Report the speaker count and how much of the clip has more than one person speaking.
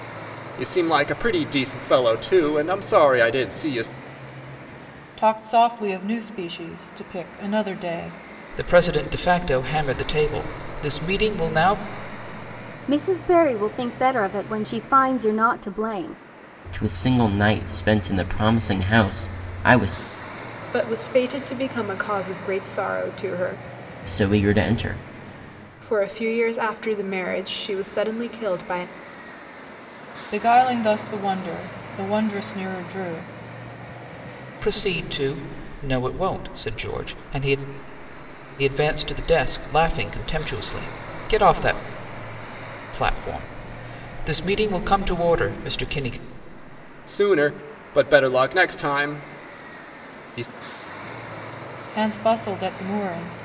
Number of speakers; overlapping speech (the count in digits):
6, no overlap